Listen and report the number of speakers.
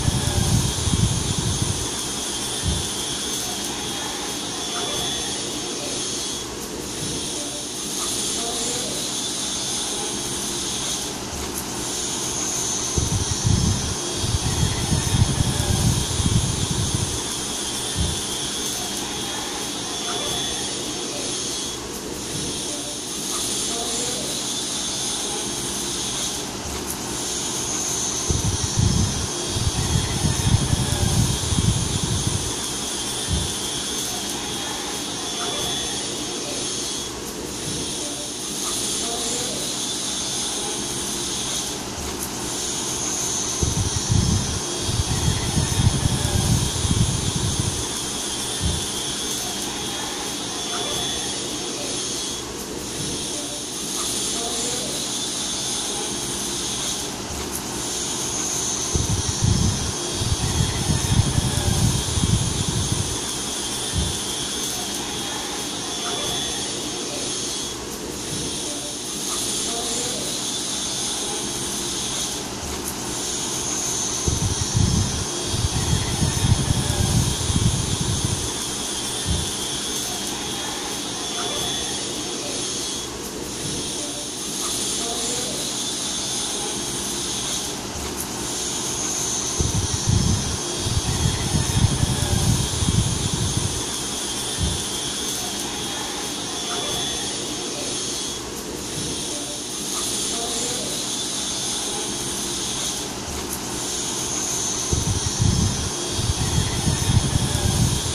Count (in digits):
0